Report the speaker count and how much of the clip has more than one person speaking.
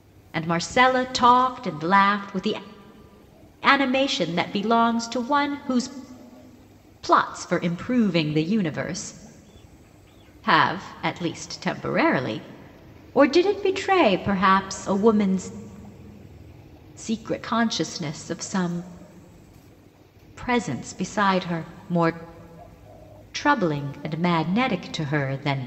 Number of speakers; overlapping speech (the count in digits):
1, no overlap